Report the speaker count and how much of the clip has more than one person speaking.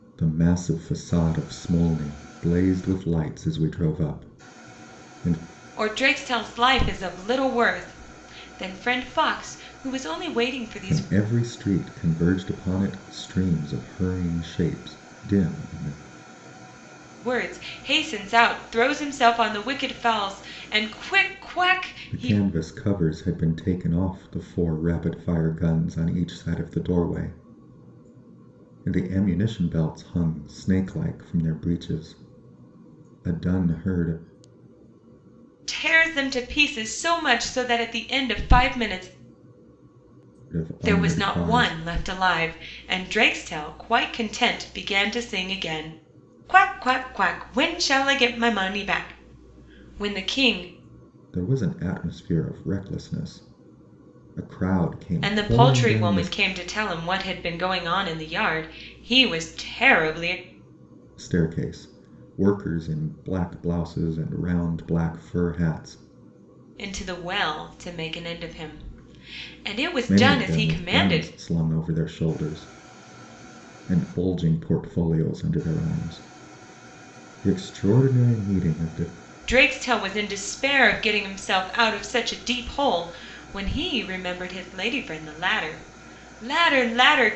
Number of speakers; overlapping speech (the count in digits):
2, about 5%